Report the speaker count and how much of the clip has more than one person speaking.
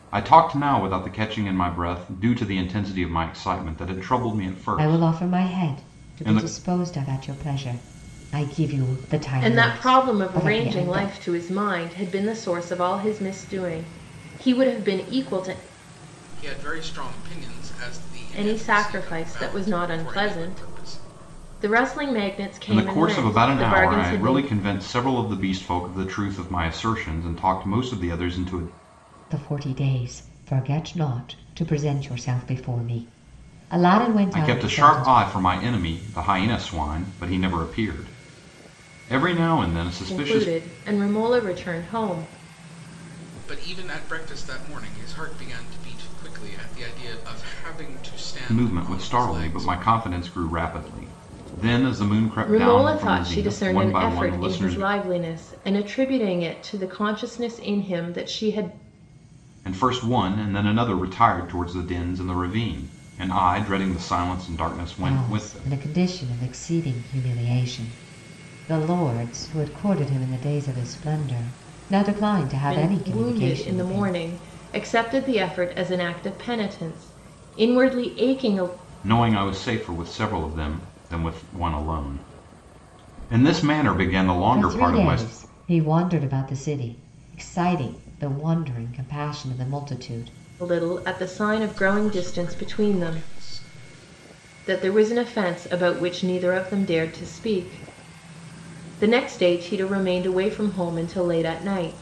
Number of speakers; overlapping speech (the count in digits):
4, about 17%